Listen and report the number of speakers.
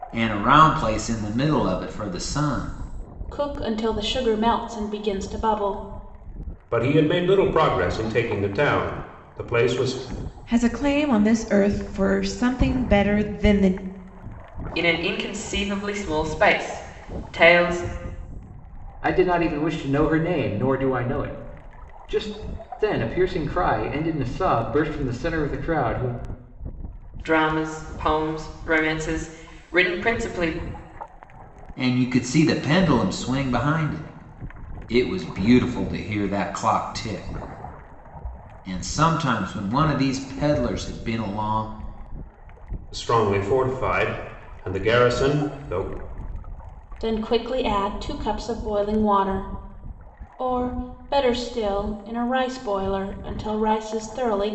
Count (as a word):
six